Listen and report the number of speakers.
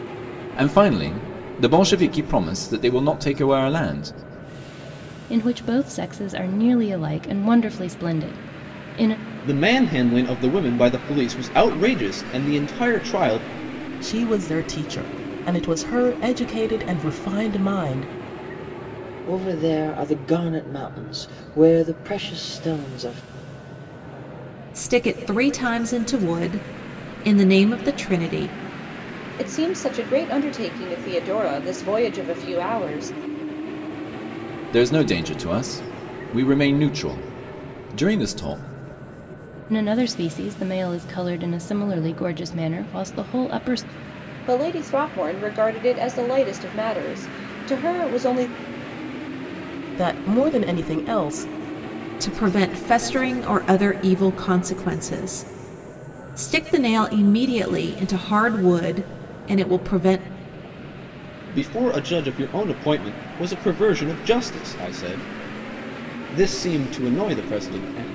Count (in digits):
7